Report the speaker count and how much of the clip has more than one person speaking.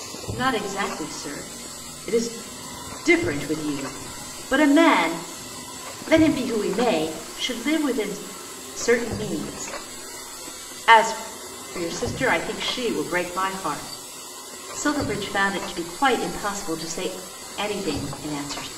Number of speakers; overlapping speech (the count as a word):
one, no overlap